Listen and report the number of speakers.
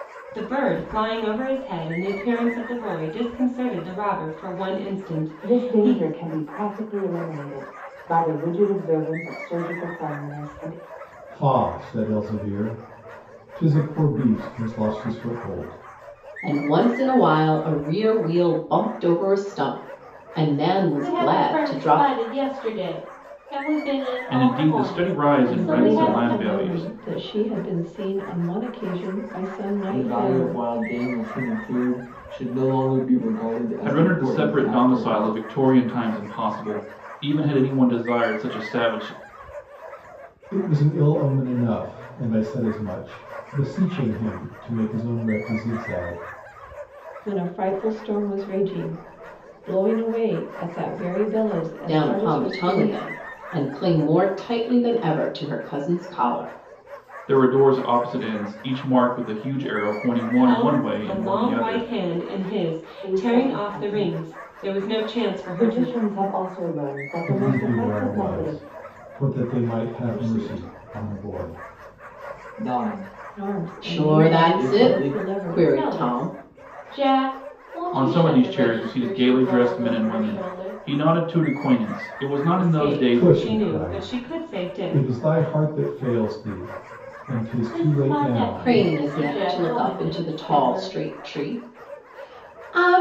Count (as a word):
eight